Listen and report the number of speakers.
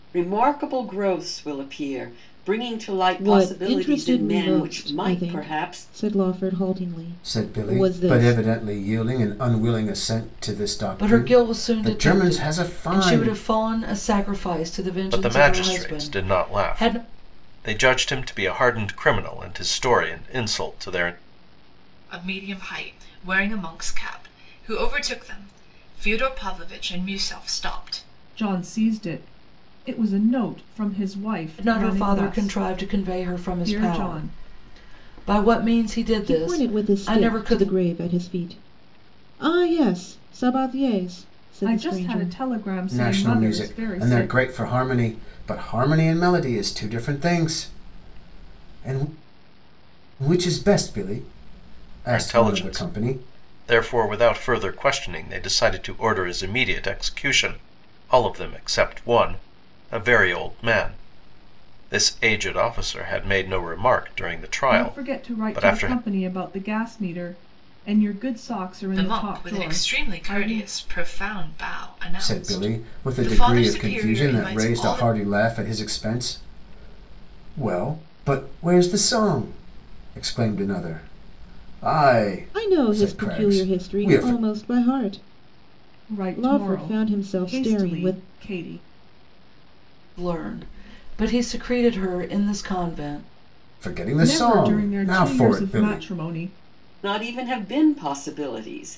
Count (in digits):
7